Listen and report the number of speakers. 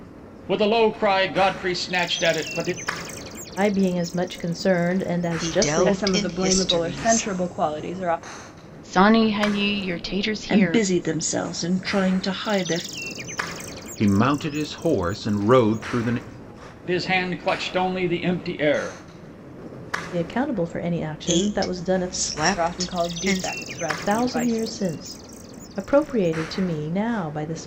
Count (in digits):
7